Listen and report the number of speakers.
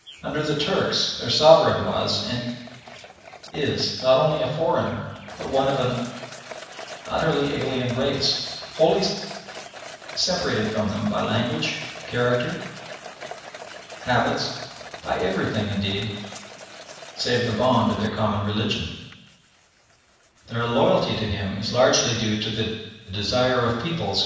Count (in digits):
1